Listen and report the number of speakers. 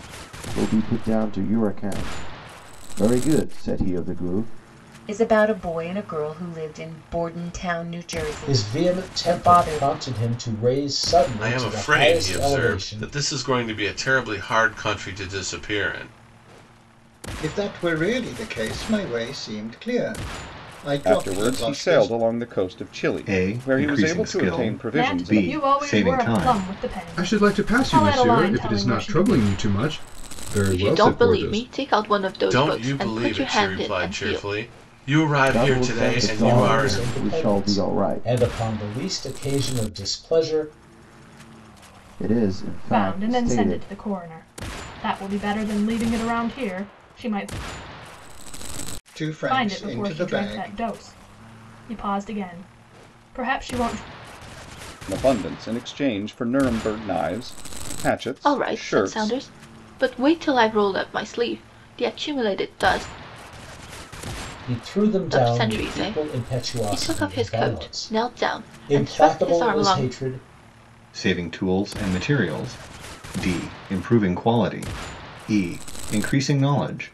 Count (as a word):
ten